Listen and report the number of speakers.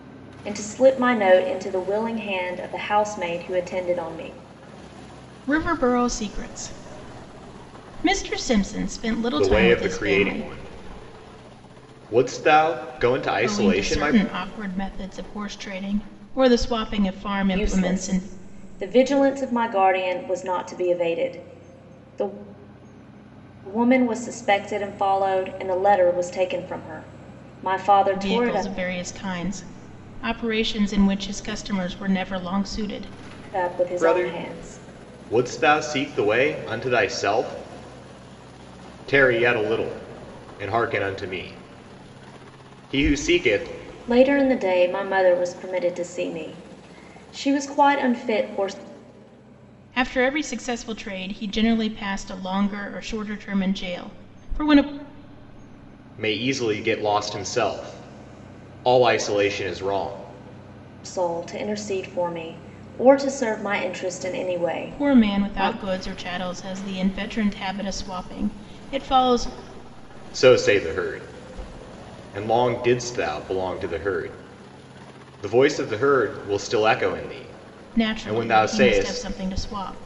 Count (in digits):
3